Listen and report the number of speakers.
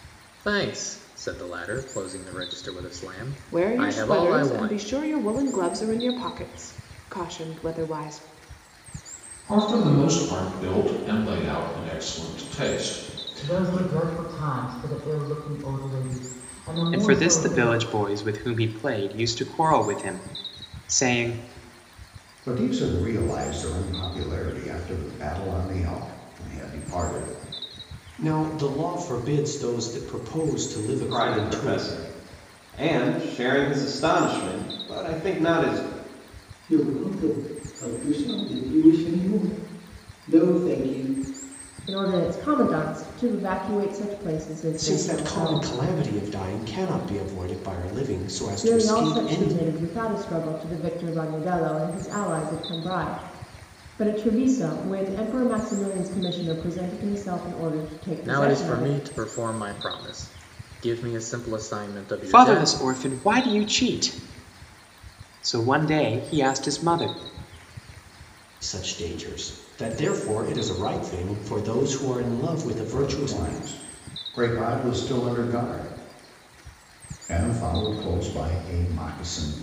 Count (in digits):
10